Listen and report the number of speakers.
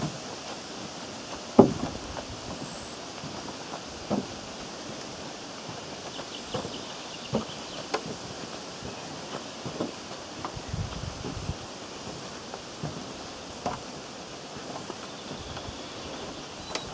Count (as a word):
zero